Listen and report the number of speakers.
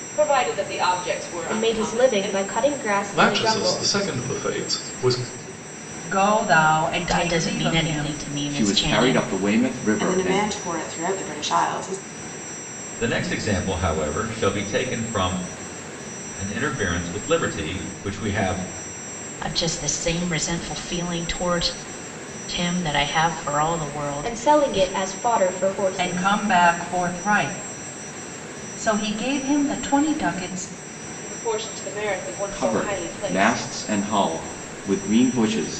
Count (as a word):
eight